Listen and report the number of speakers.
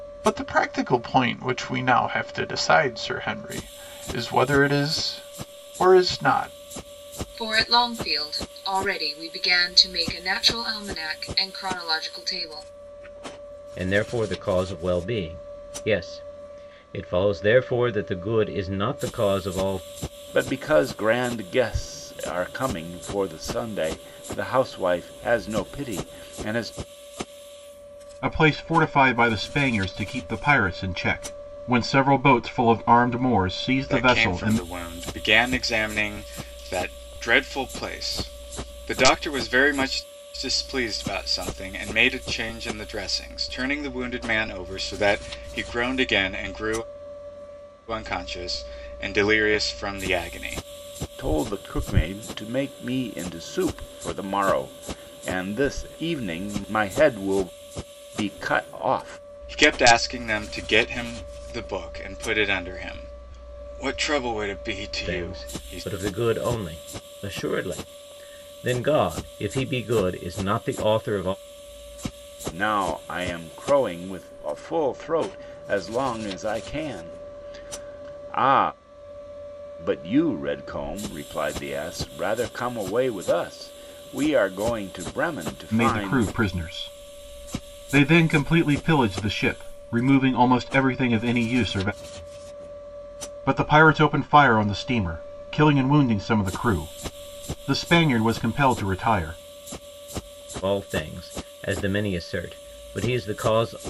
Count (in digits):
6